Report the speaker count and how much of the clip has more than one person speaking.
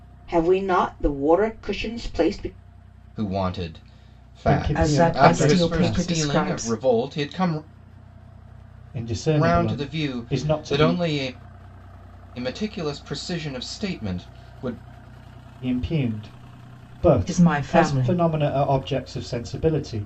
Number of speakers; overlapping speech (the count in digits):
4, about 25%